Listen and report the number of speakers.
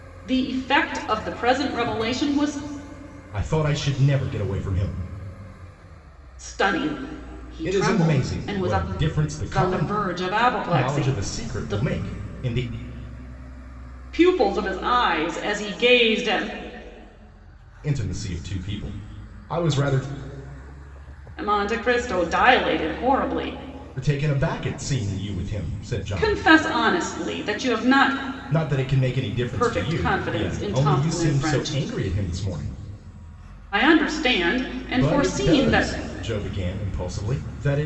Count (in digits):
2